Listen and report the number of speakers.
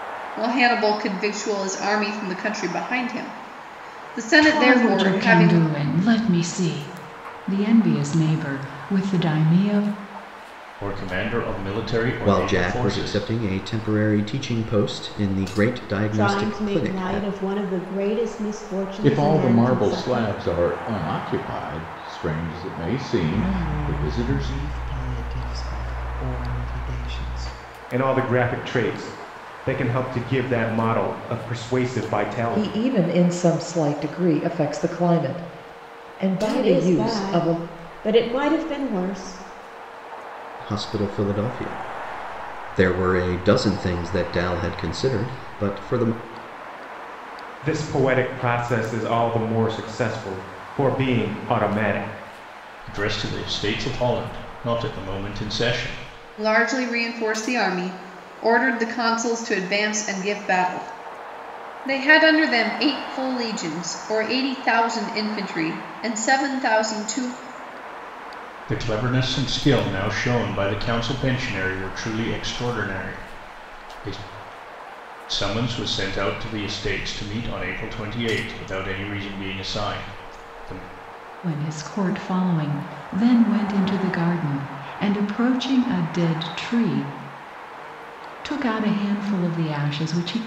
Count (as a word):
nine